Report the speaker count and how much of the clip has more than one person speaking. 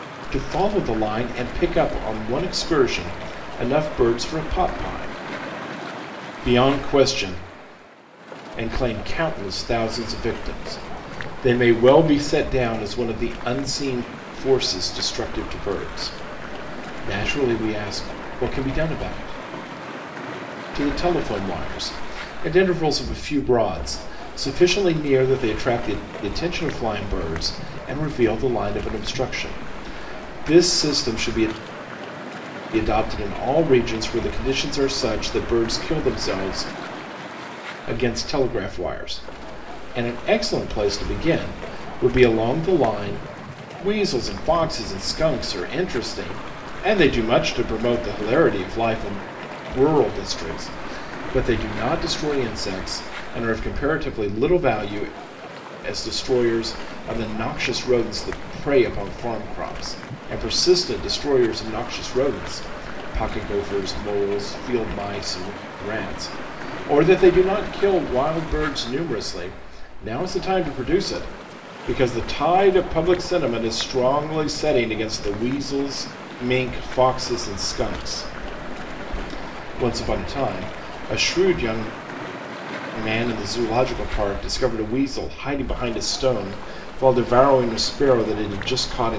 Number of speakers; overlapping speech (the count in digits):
1, no overlap